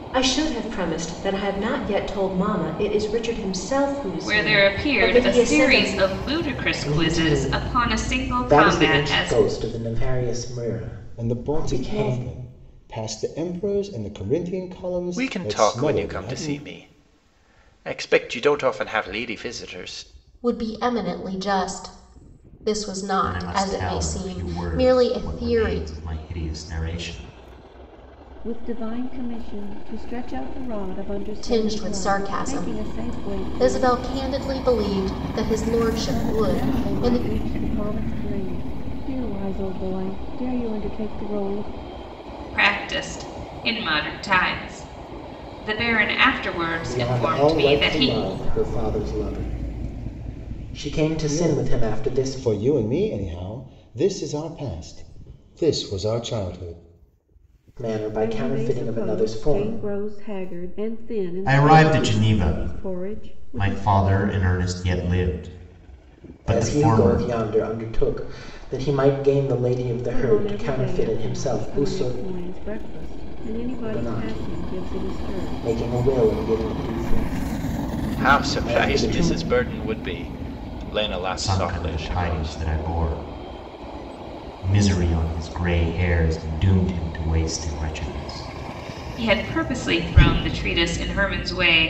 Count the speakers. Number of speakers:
8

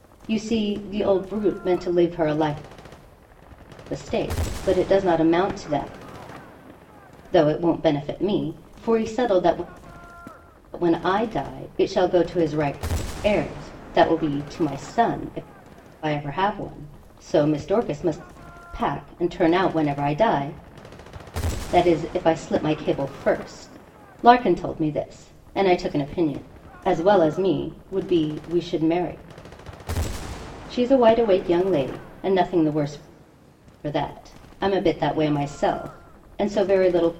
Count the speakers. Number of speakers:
1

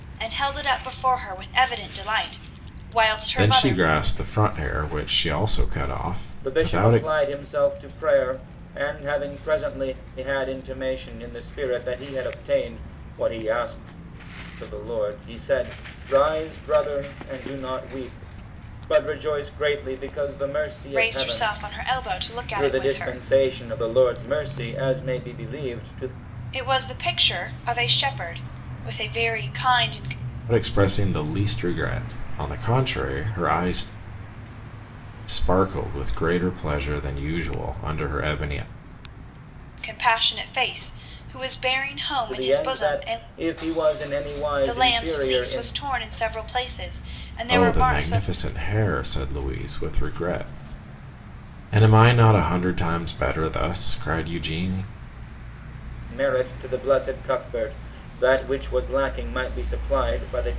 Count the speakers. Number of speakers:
3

